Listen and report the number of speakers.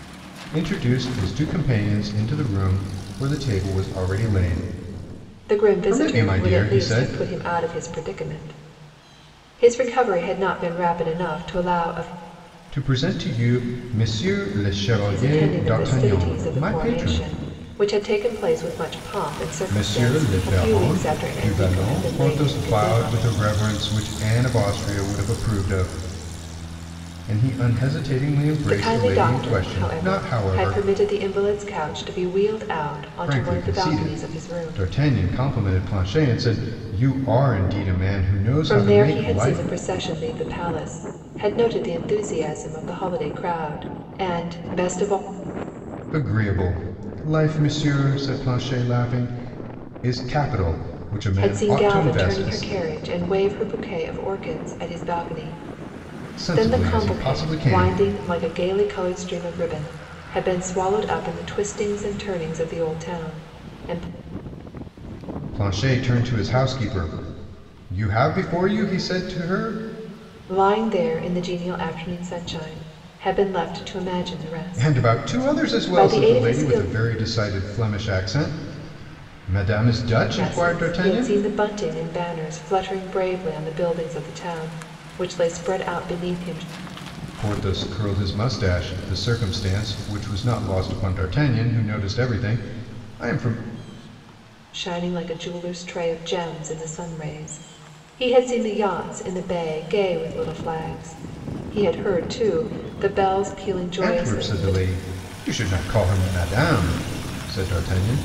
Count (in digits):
2